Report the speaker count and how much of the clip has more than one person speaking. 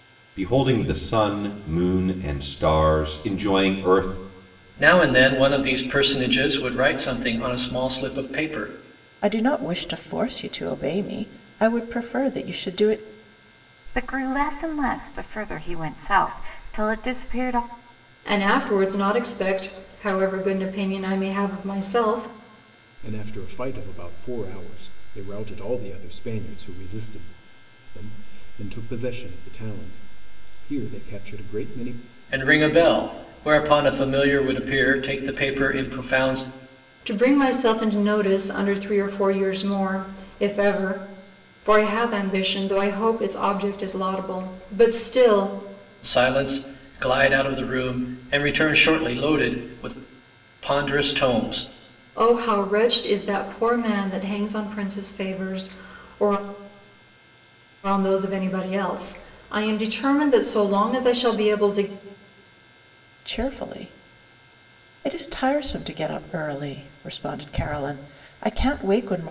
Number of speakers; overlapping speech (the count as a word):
six, no overlap